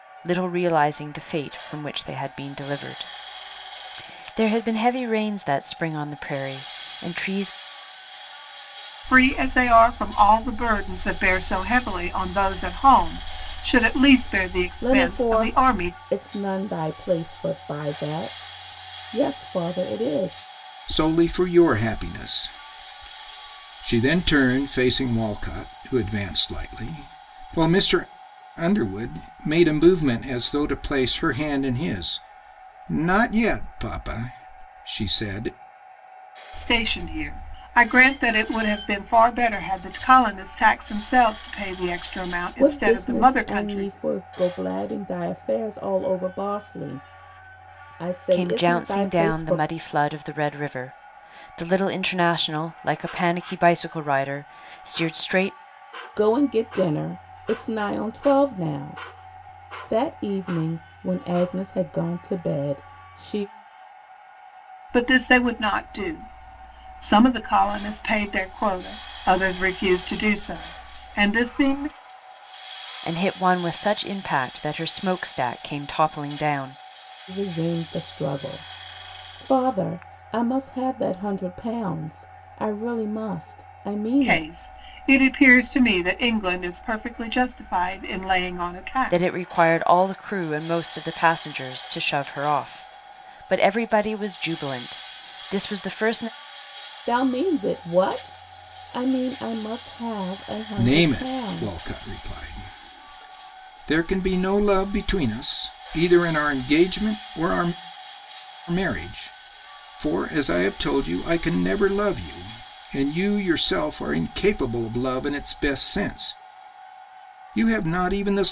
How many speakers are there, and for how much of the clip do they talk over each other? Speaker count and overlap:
four, about 5%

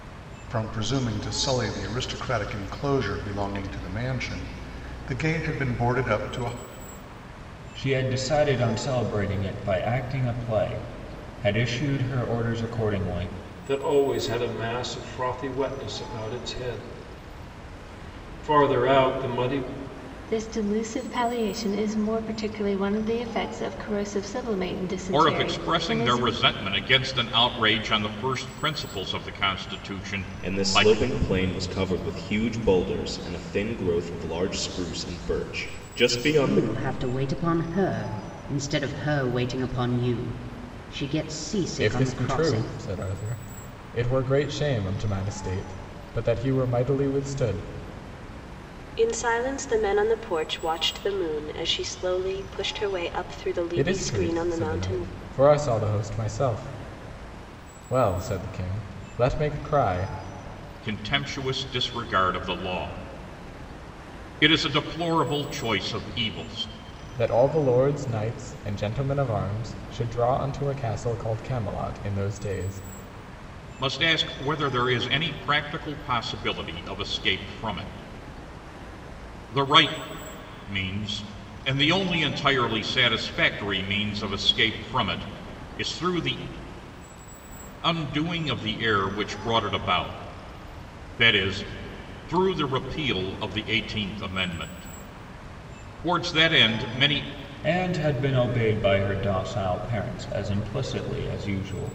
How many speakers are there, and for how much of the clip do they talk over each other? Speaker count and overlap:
nine, about 4%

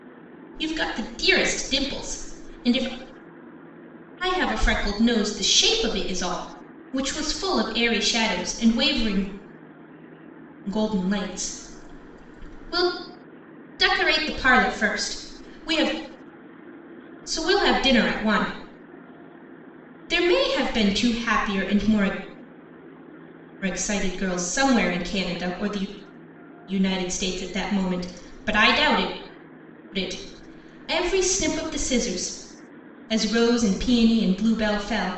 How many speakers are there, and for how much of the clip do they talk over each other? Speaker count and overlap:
one, no overlap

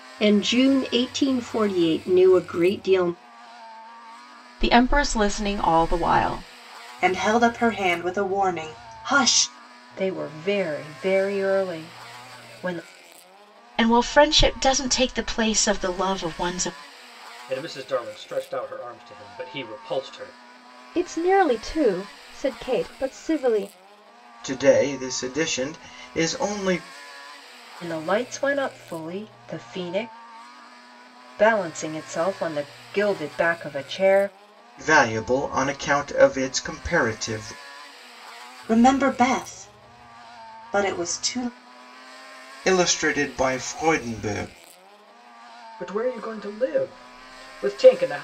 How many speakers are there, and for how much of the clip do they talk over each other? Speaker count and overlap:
eight, no overlap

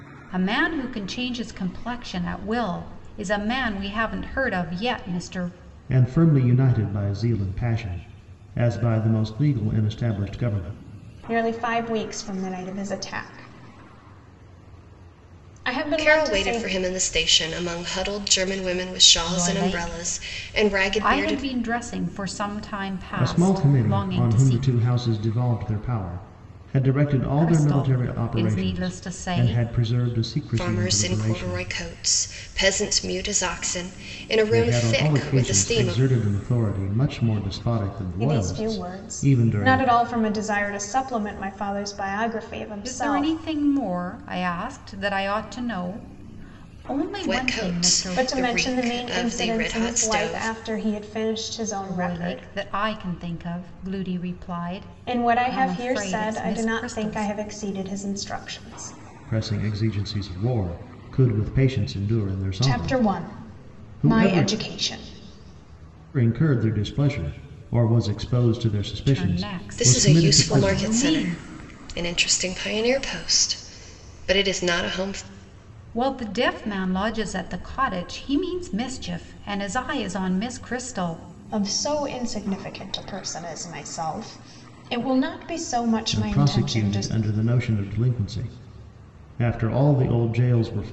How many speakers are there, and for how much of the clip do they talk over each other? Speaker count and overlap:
four, about 26%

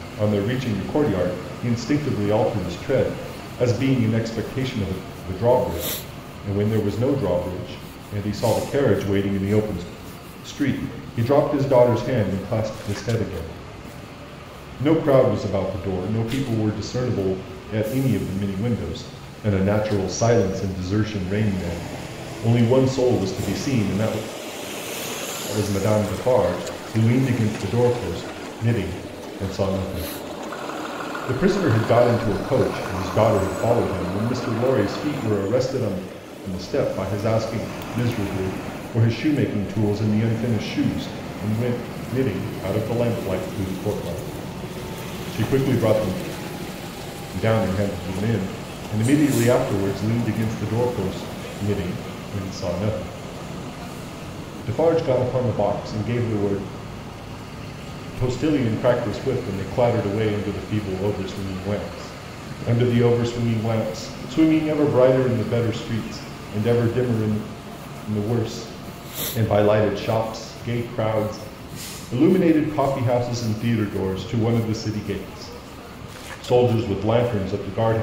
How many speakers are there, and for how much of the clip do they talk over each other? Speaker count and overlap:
one, no overlap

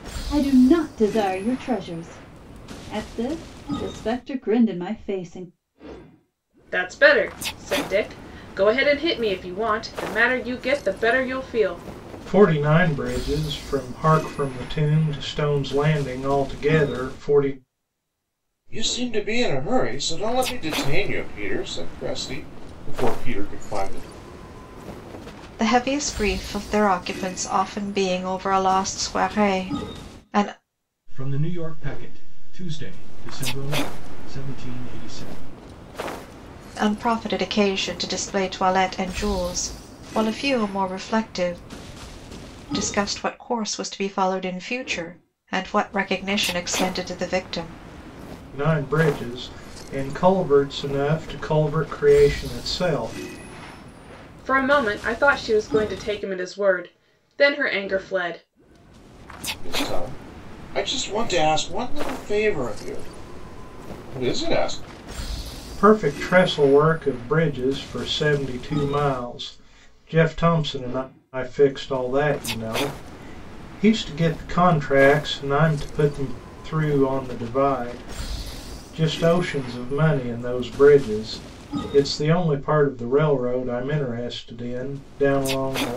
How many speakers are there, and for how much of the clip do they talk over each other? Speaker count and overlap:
six, no overlap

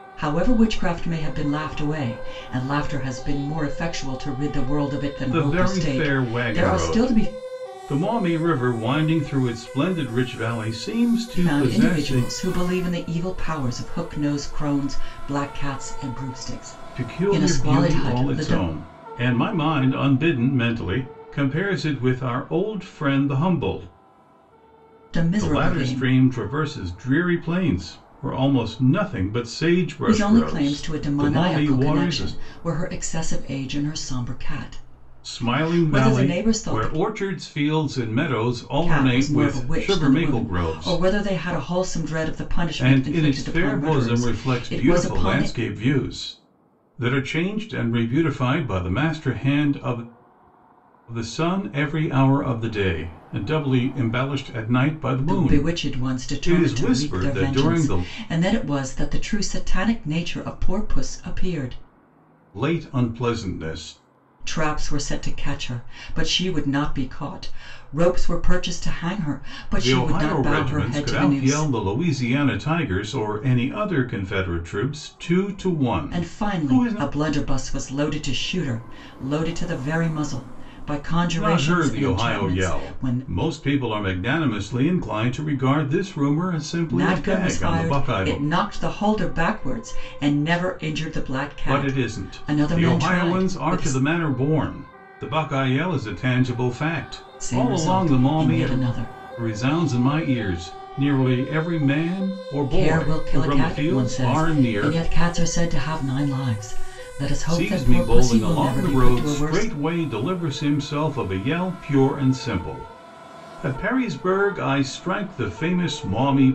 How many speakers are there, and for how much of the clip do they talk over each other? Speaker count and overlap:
two, about 28%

